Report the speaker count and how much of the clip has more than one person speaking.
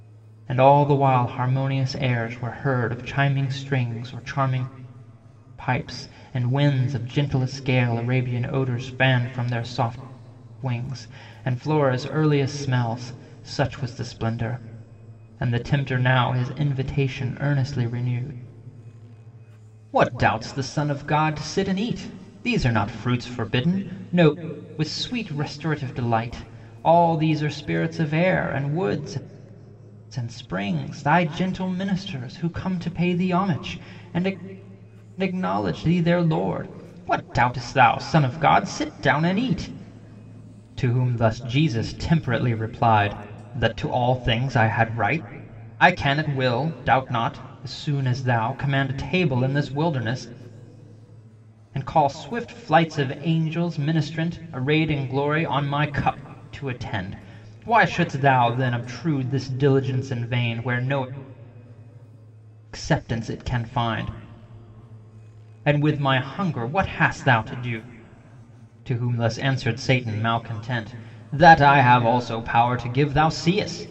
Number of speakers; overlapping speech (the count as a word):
one, no overlap